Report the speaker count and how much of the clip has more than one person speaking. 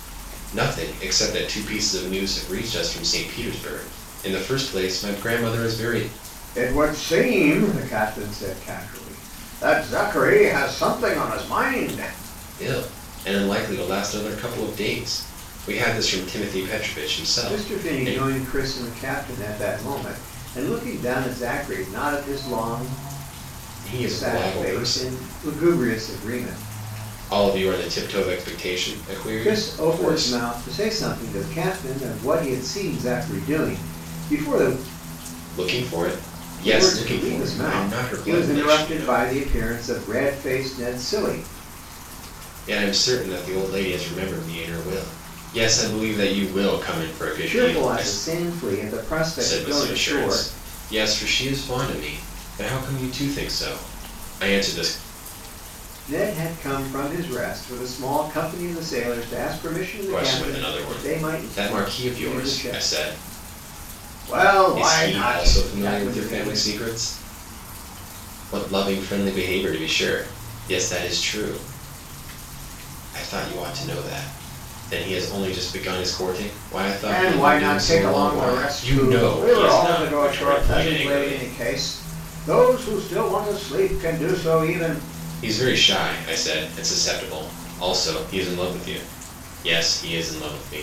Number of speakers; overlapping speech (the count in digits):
2, about 18%